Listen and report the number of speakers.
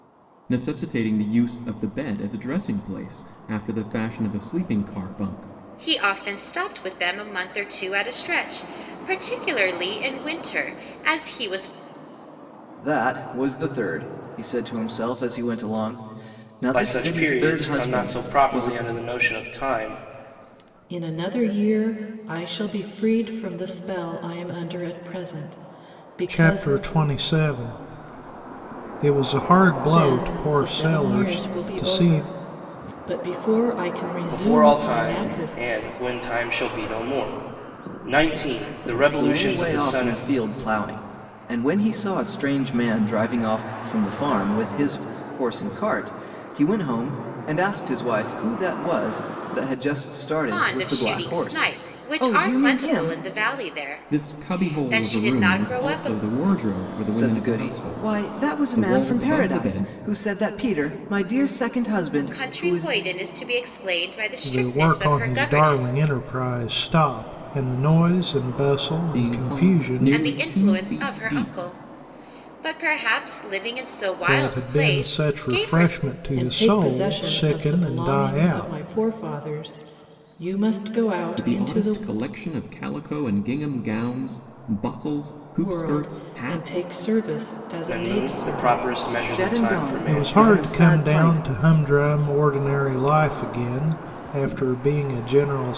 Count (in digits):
6